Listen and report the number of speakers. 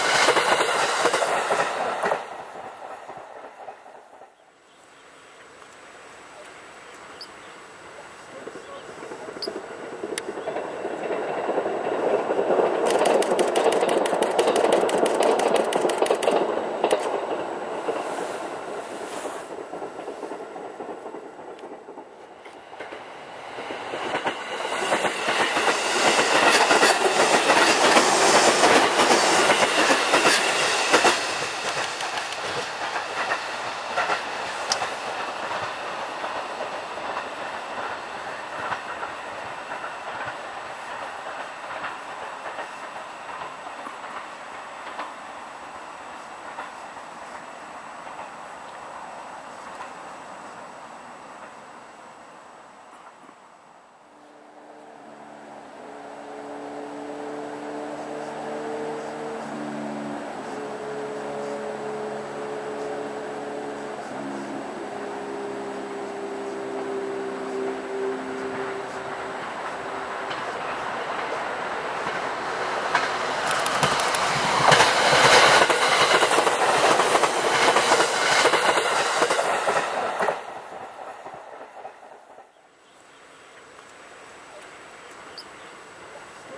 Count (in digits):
0